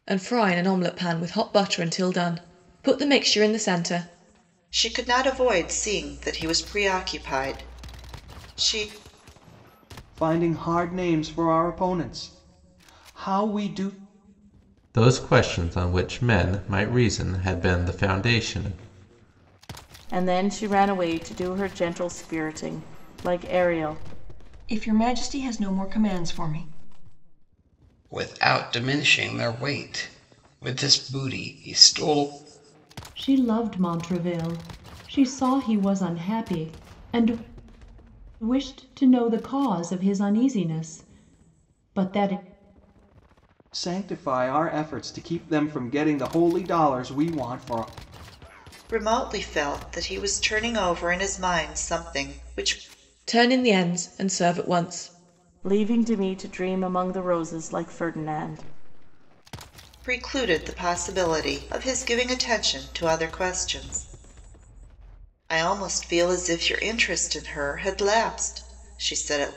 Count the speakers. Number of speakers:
eight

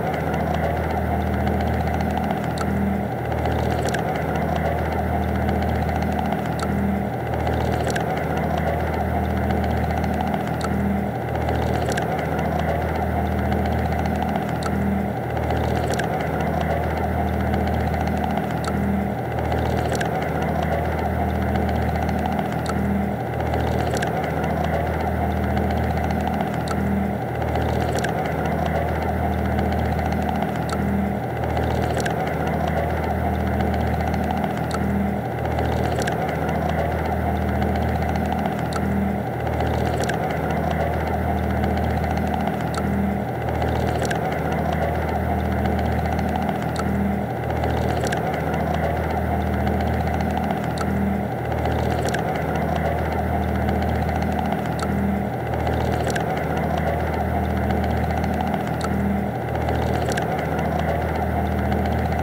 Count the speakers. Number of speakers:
zero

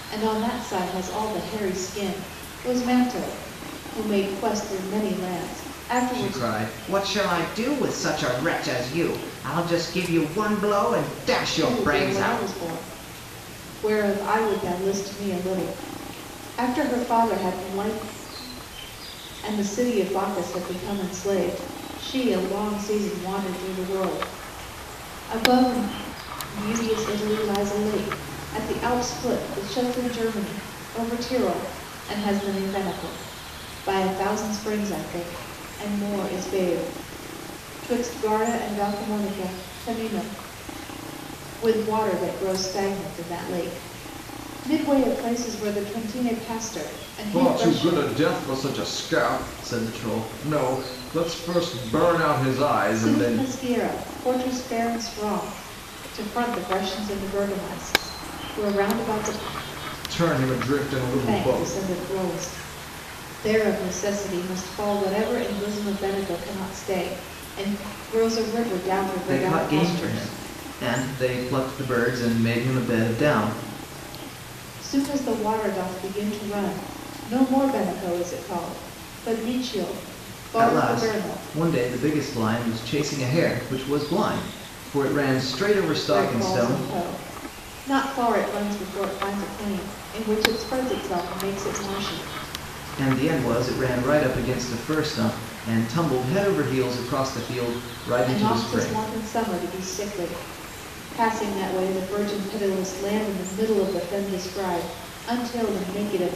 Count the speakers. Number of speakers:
two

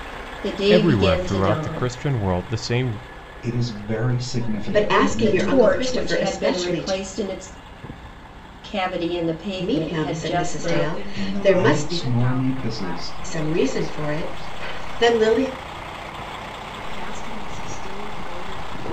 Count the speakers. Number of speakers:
five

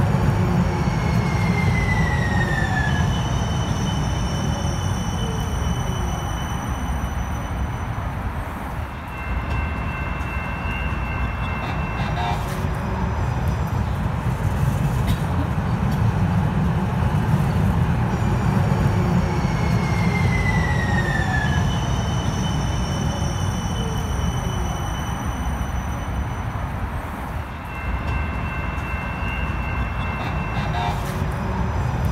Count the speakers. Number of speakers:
zero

